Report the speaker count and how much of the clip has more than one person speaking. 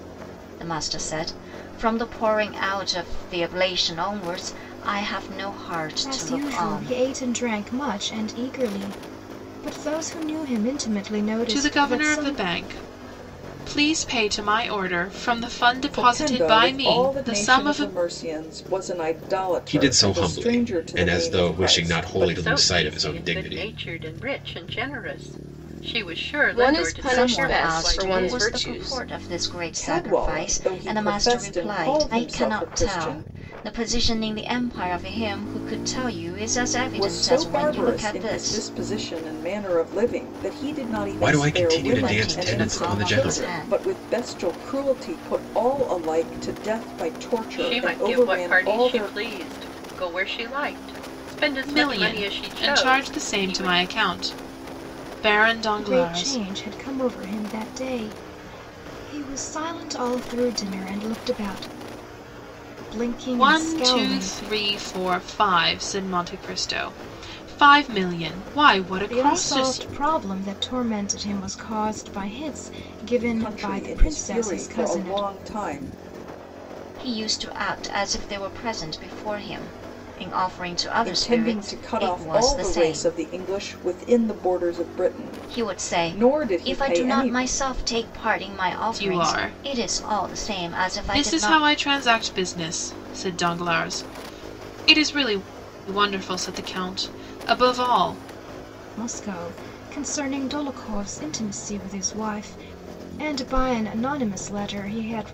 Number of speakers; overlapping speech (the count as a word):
seven, about 32%